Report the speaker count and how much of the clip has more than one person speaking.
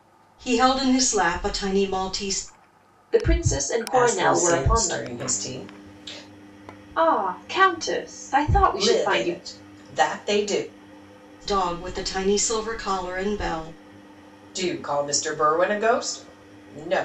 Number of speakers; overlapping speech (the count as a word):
three, about 11%